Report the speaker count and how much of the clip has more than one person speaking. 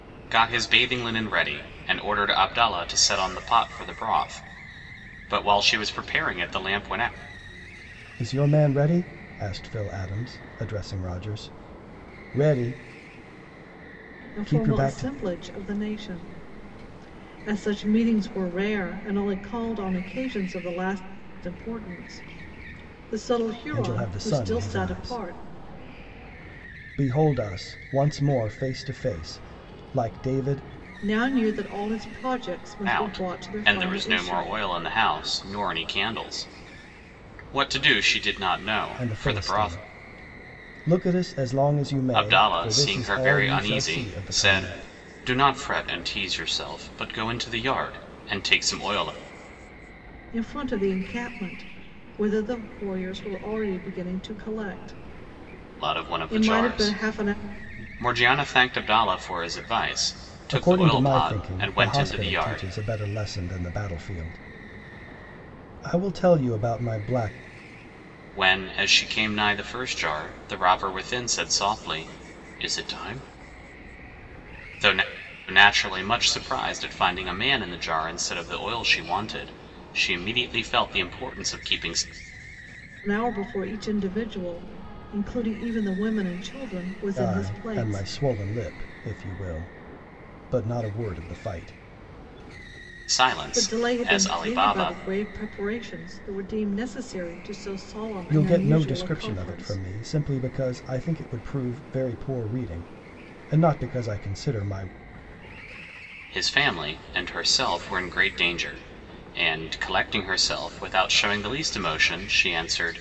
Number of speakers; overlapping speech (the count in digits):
3, about 14%